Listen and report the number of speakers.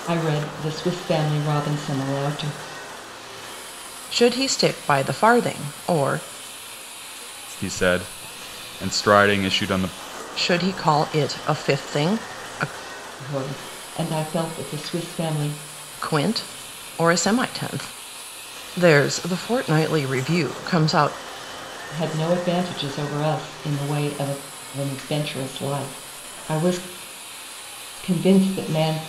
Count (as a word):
three